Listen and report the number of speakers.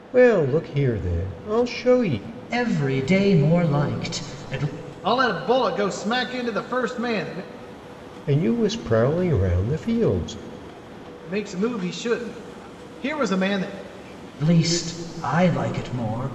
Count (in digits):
3